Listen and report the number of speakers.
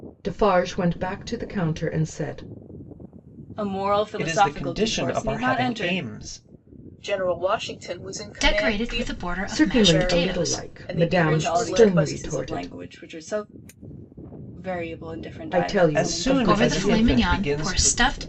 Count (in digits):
5